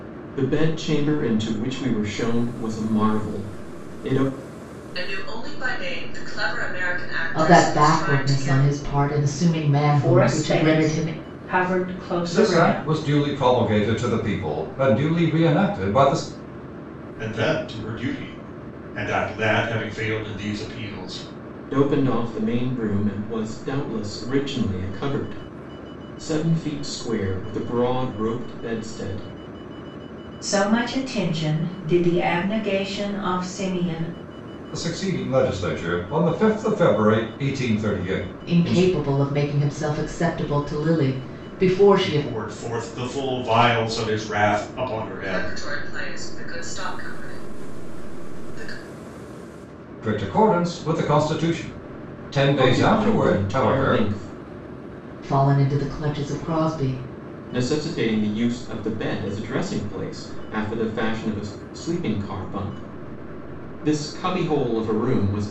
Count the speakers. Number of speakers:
six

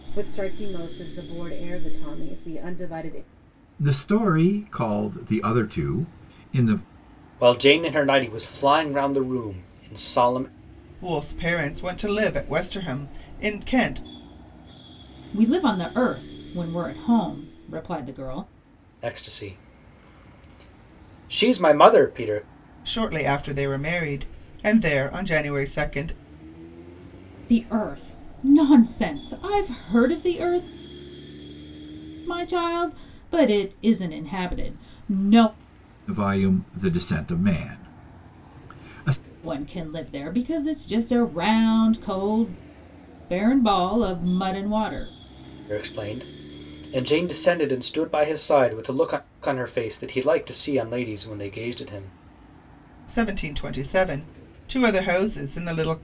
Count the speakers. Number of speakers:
five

